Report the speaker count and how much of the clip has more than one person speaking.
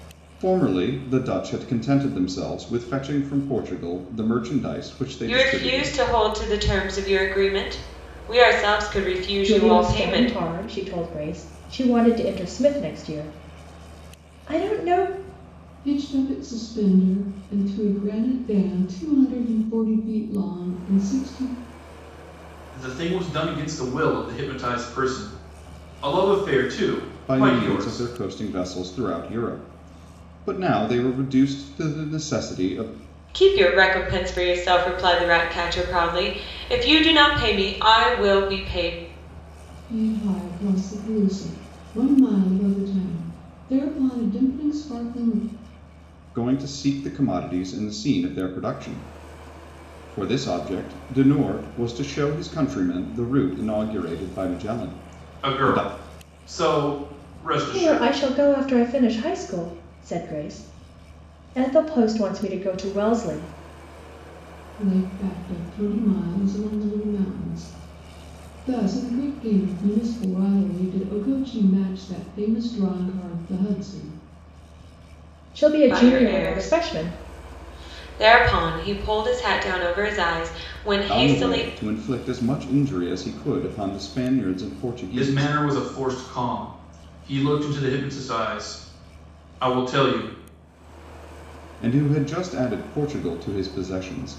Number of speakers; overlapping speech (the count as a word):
five, about 6%